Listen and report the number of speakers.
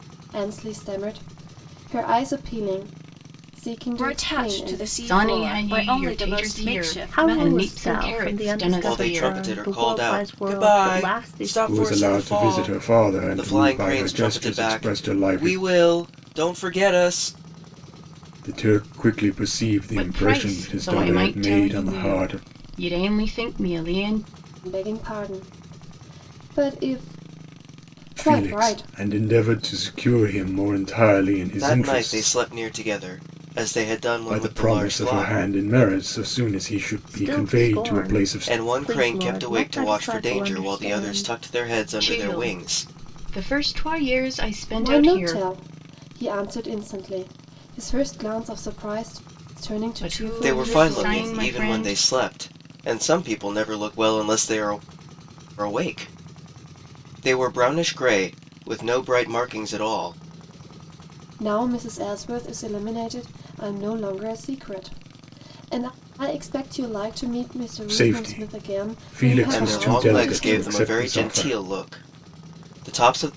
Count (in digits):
6